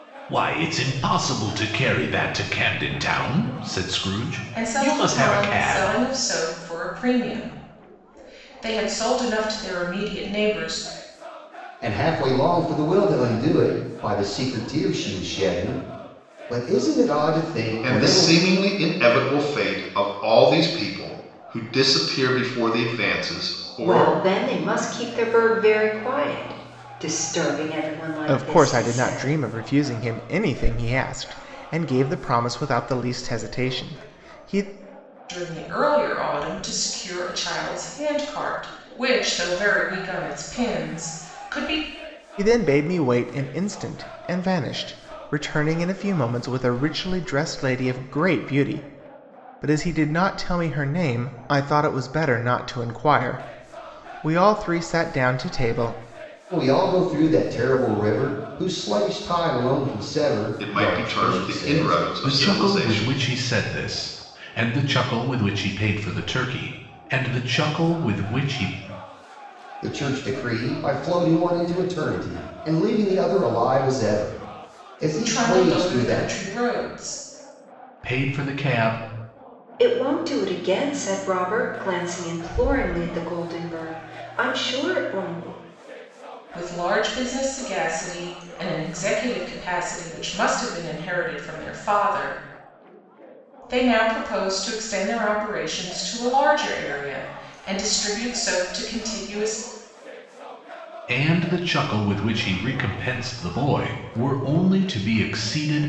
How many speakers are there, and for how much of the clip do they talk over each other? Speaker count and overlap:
6, about 7%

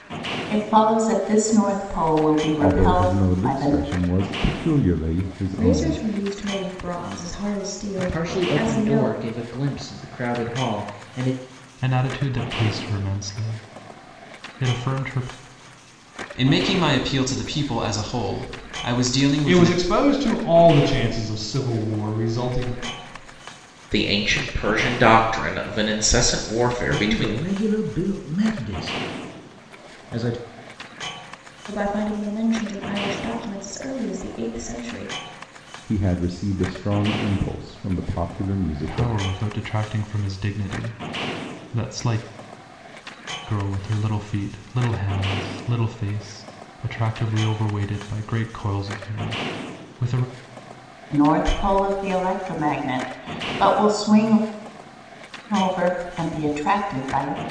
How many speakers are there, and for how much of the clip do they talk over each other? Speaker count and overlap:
9, about 7%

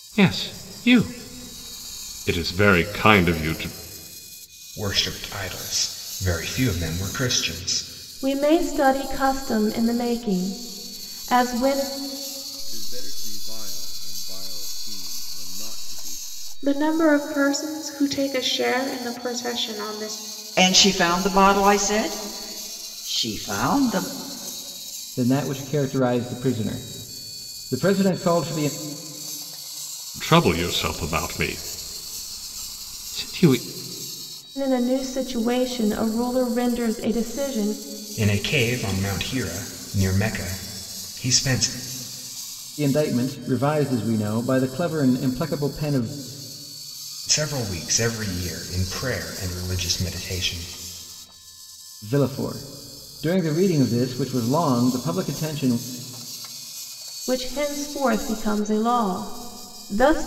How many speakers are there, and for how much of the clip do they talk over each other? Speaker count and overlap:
7, no overlap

